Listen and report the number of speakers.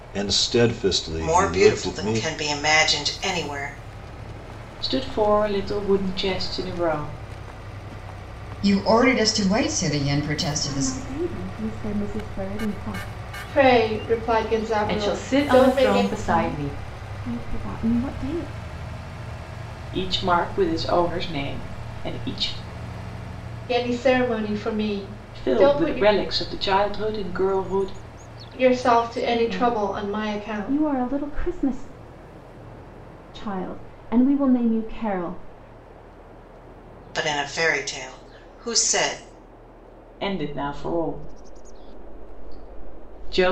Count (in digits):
7